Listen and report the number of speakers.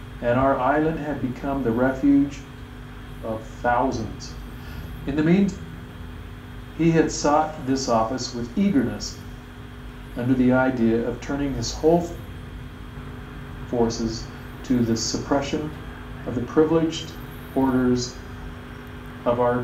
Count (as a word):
one